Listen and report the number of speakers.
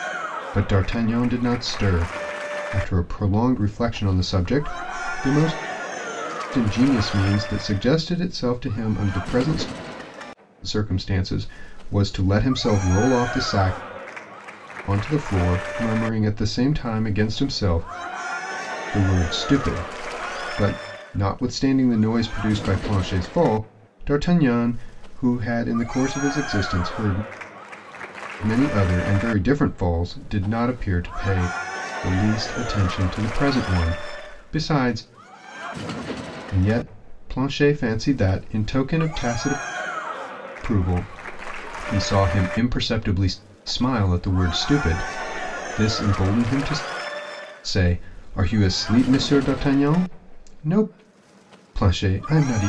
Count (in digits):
1